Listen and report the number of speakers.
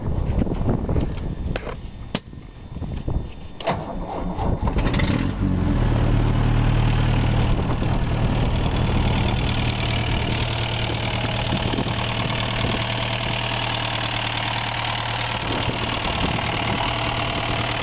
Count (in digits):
0